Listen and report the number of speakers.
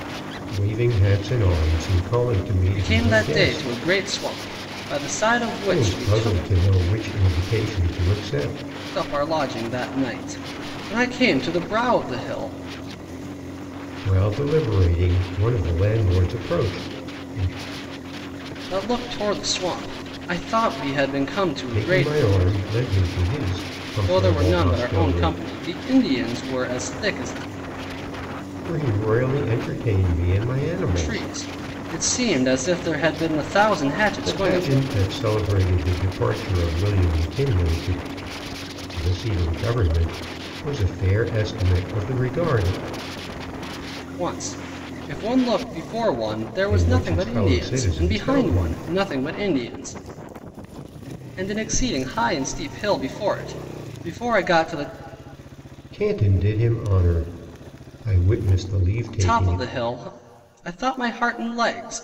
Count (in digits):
2